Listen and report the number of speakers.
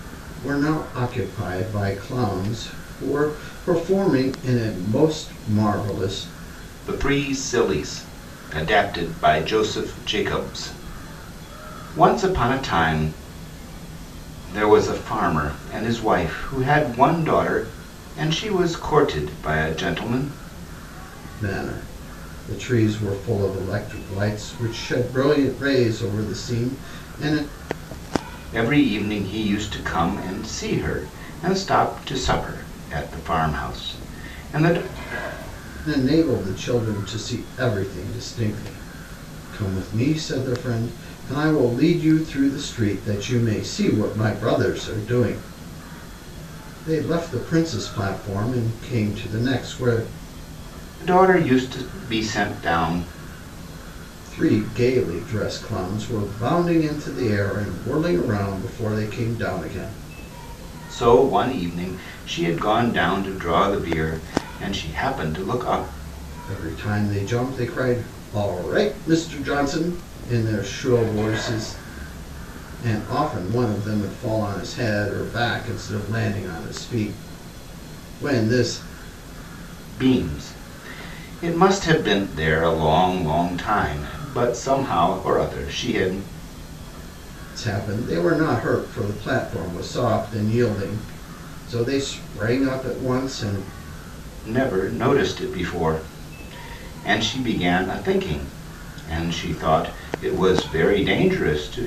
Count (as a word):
two